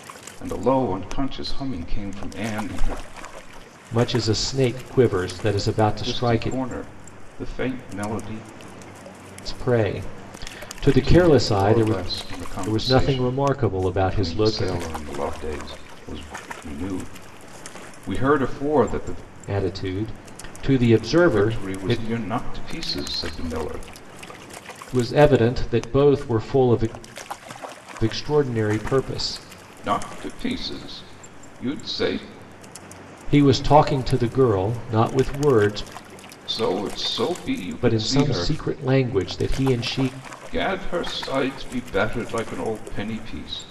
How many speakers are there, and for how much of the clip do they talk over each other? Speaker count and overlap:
two, about 11%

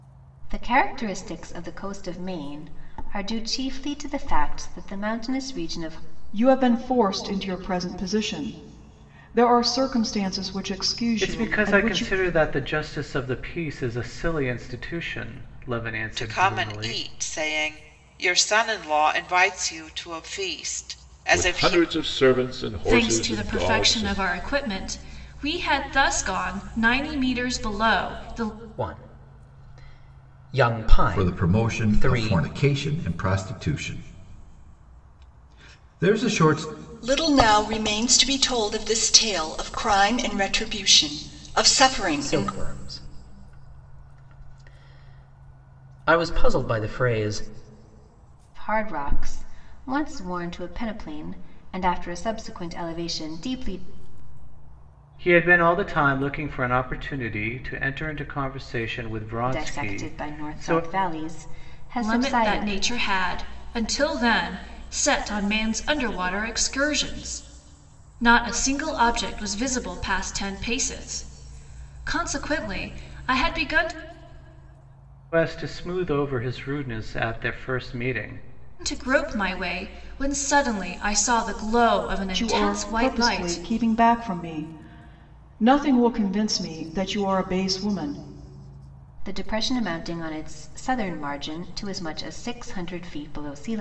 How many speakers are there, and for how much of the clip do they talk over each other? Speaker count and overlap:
nine, about 10%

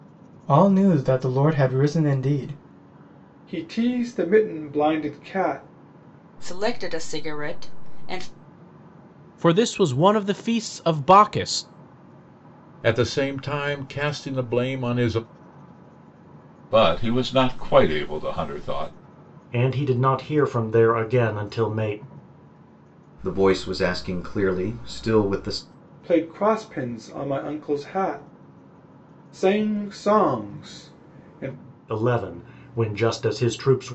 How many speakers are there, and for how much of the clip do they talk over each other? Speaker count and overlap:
eight, no overlap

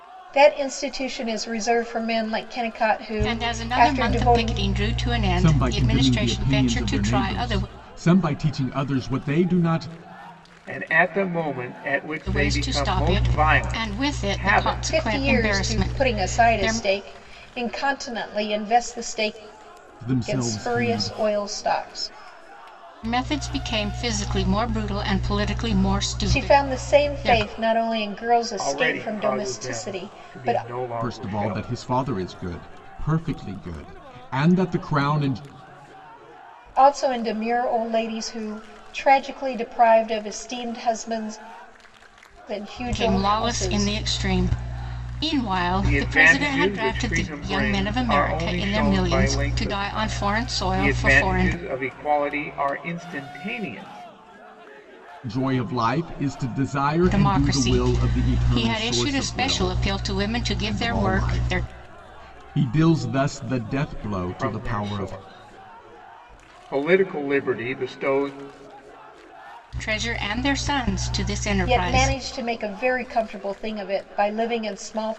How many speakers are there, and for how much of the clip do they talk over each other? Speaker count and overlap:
four, about 34%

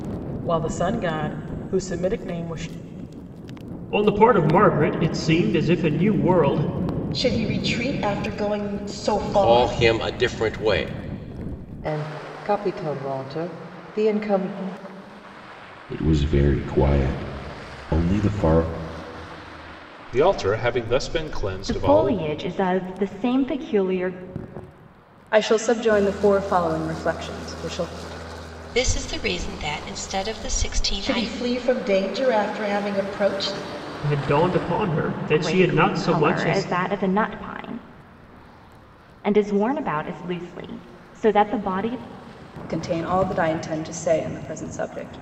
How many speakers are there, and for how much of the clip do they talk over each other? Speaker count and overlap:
ten, about 6%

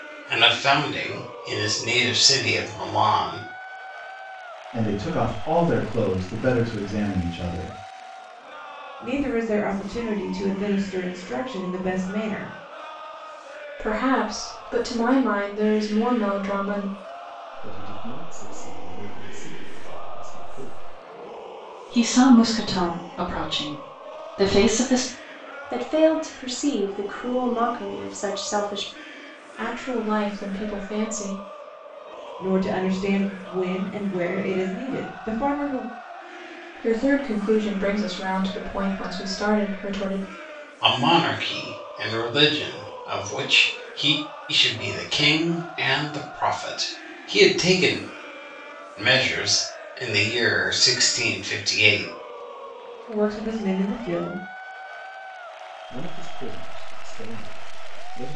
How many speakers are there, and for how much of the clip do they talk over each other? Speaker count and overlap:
seven, no overlap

